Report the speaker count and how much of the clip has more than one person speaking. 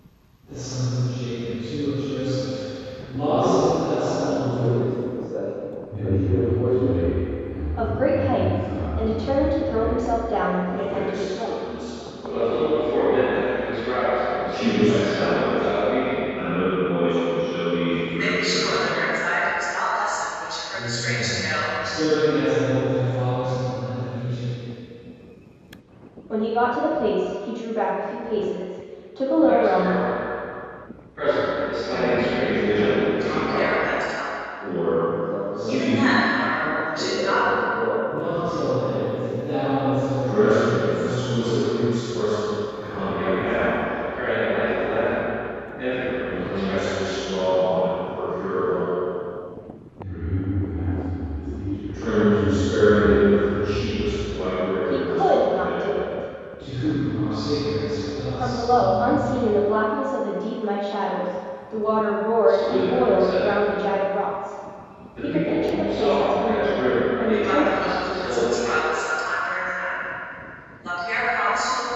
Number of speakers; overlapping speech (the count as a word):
eight, about 49%